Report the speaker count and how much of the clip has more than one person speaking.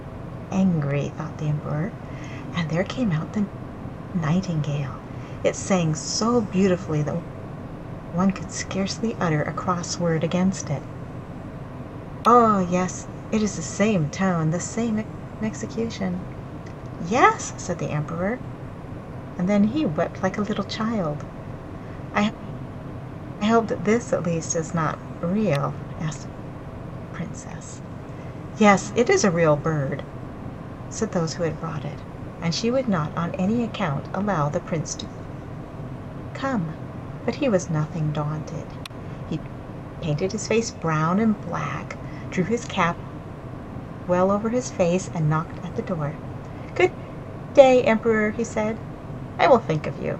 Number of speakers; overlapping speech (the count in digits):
1, no overlap